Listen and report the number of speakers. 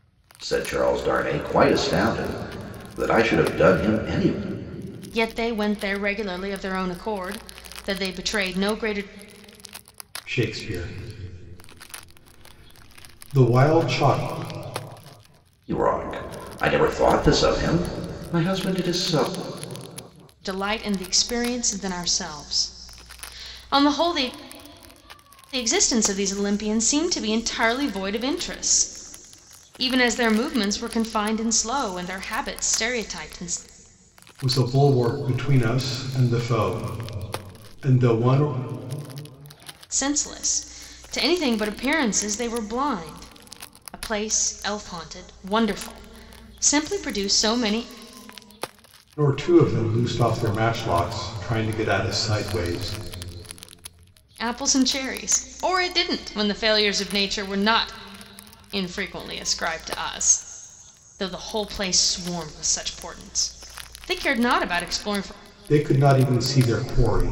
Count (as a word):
three